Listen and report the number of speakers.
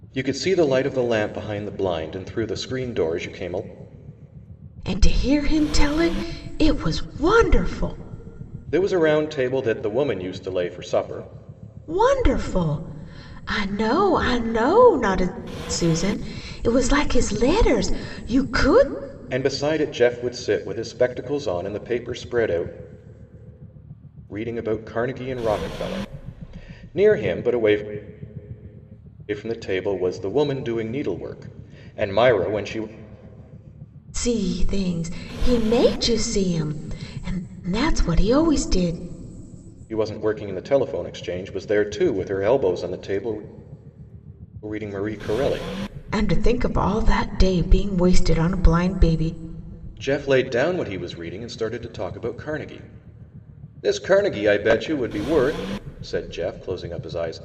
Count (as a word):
two